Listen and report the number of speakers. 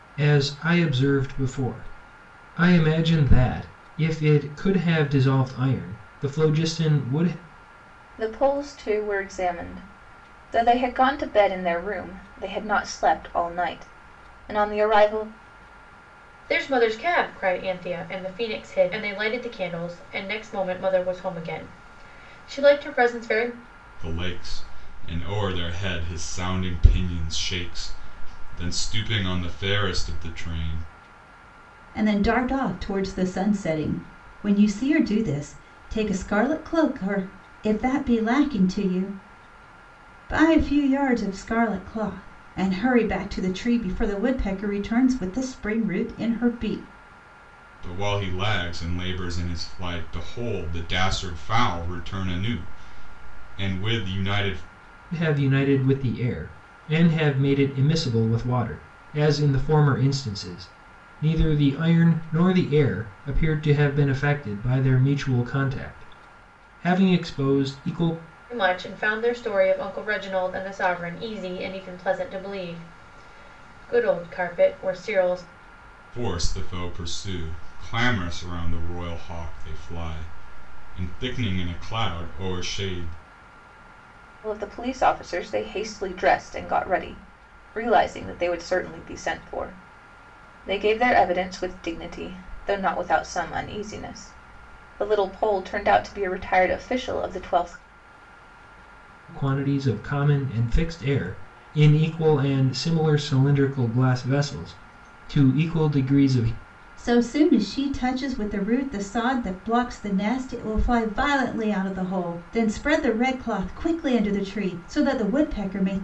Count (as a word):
five